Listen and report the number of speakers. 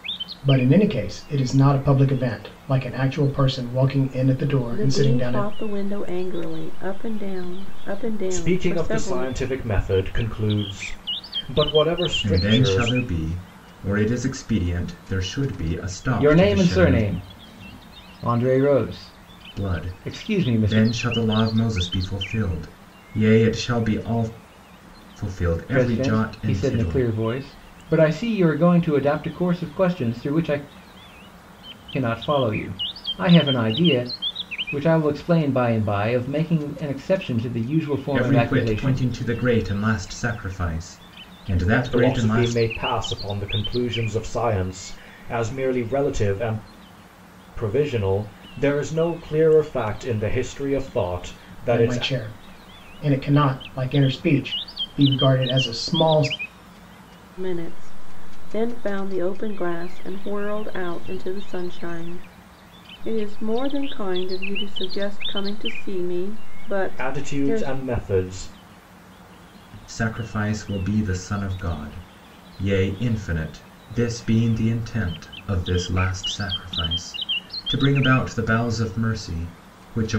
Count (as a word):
five